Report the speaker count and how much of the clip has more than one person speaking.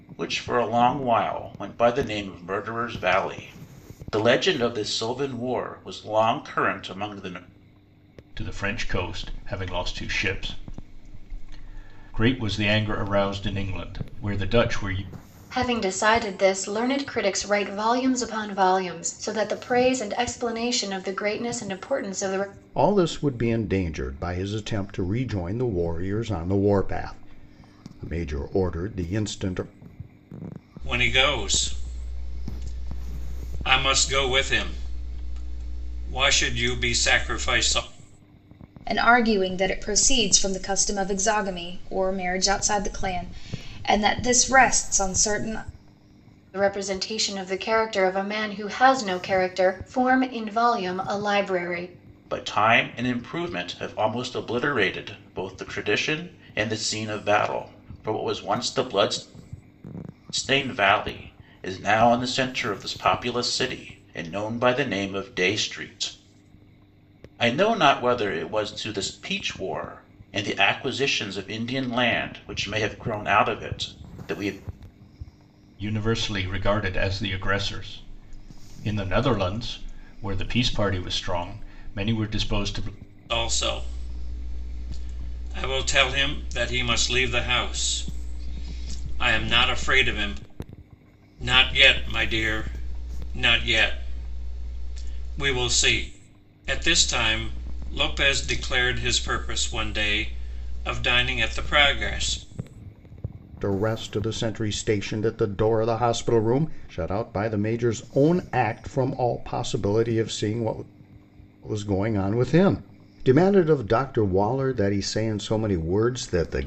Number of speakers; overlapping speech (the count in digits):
6, no overlap